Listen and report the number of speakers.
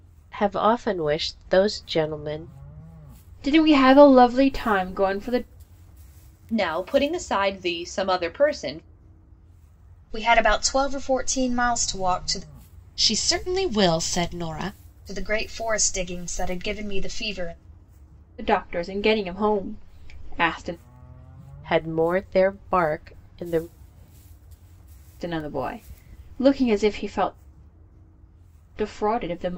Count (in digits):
5